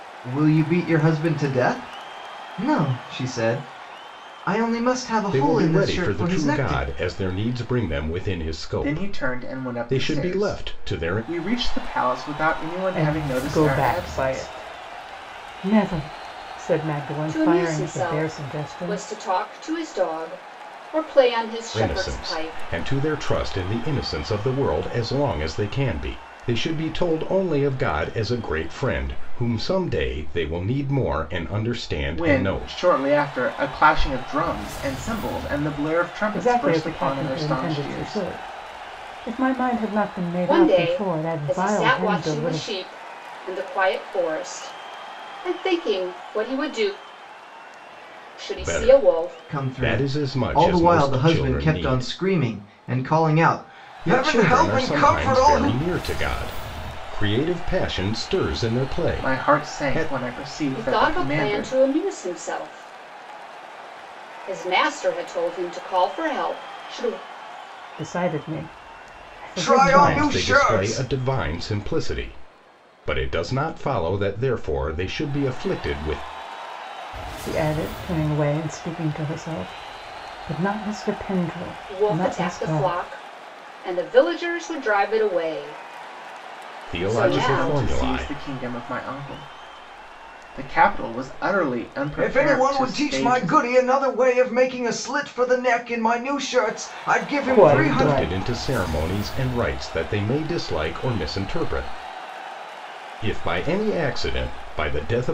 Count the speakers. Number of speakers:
5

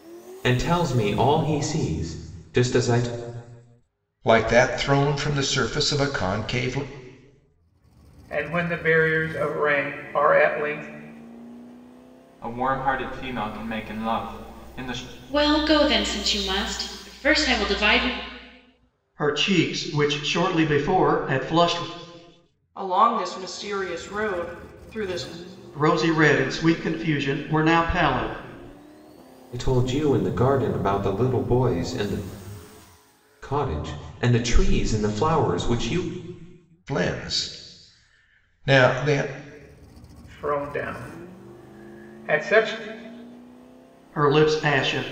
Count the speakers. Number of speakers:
7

